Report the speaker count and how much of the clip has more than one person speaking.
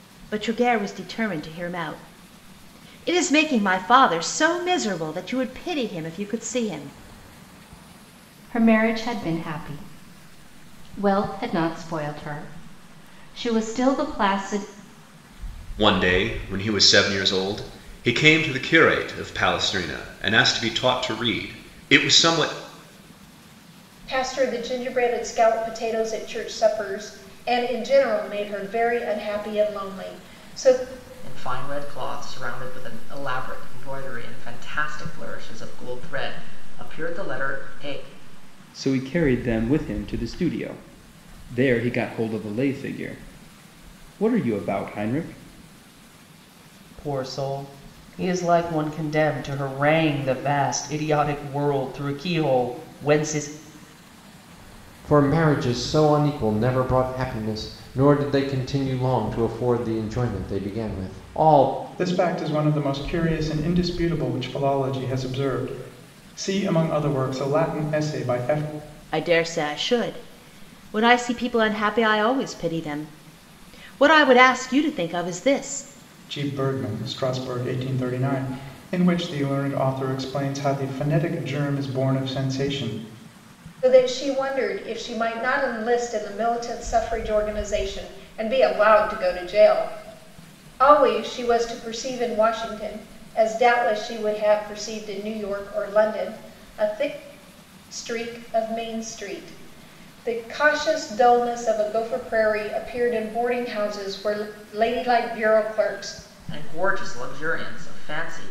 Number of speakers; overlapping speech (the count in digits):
9, no overlap